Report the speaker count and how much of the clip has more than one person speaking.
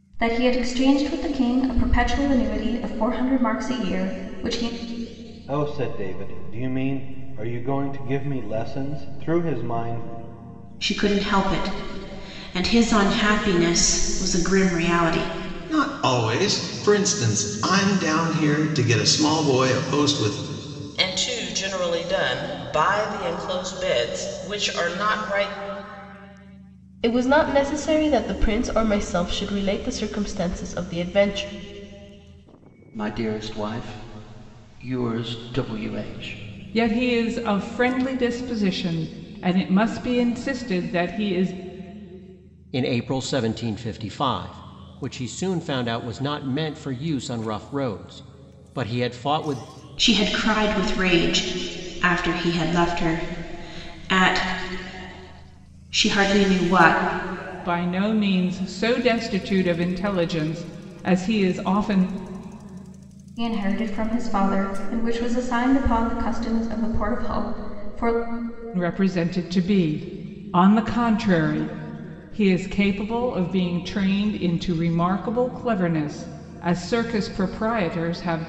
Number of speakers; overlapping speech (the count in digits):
9, no overlap